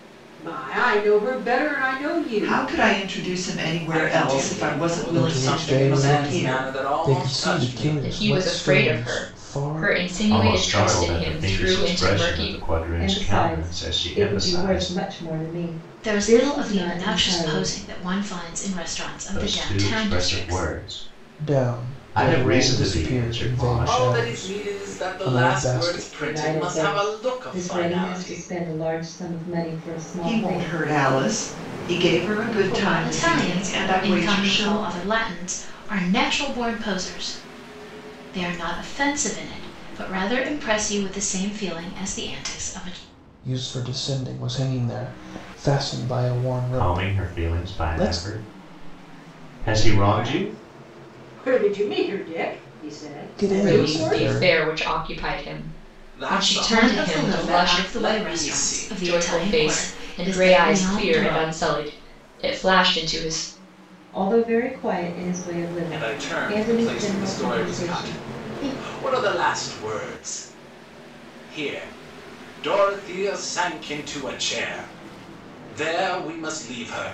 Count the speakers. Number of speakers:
eight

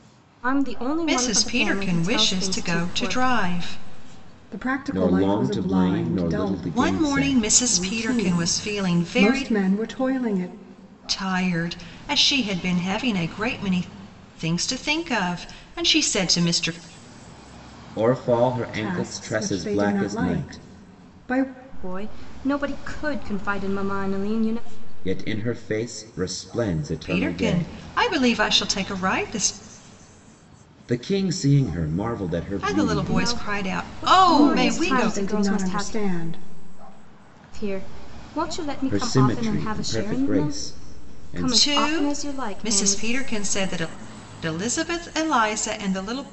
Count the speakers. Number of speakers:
four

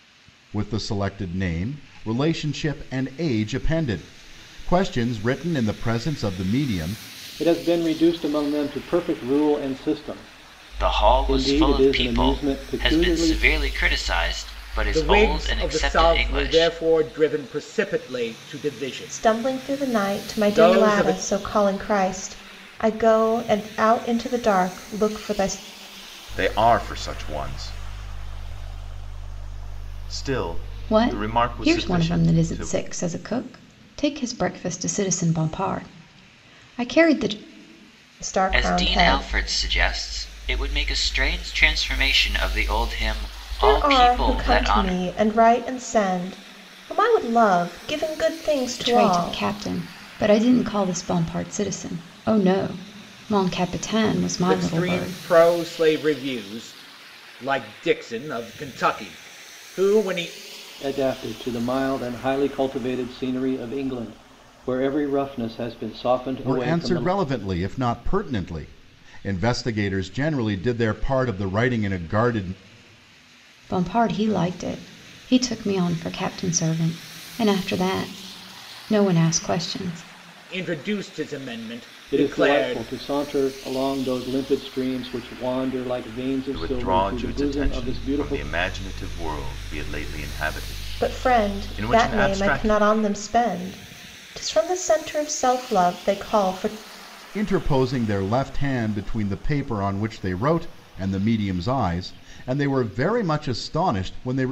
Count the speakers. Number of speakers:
seven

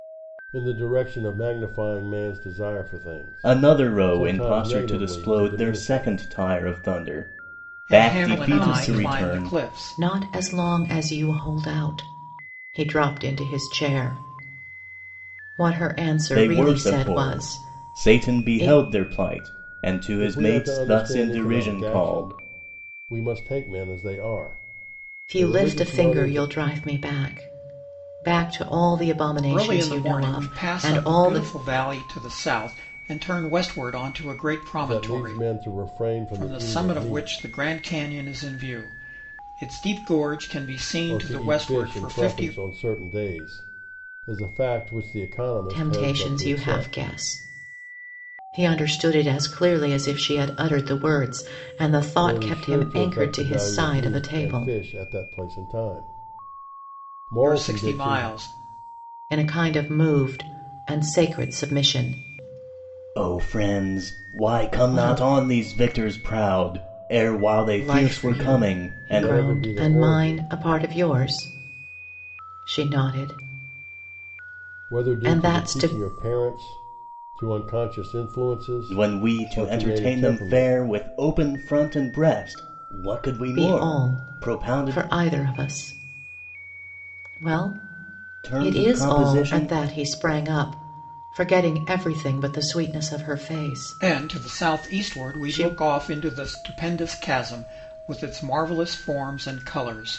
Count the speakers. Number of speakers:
four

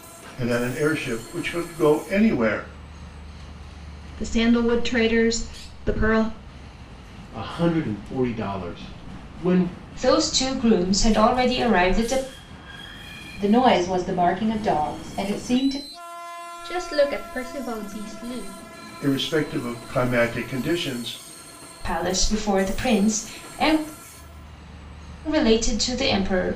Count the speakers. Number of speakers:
six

